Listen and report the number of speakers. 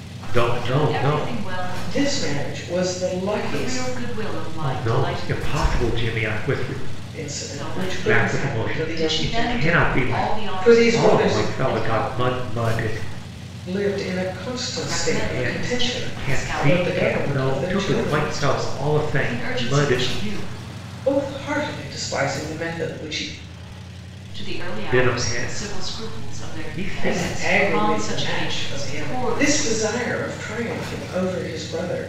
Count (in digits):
3